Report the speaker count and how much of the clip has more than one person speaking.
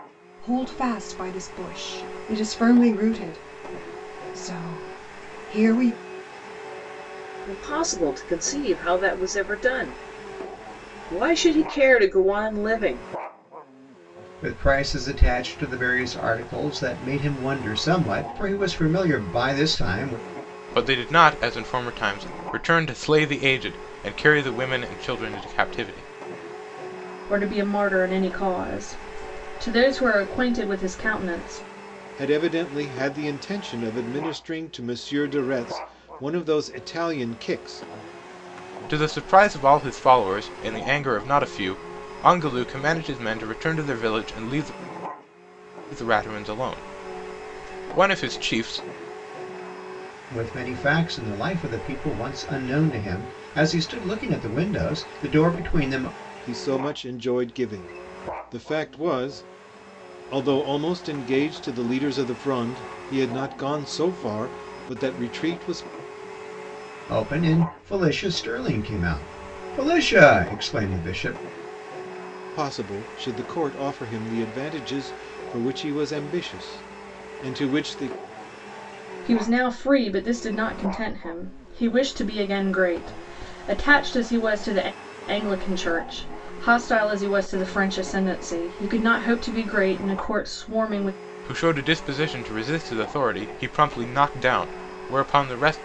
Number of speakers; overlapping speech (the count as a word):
six, no overlap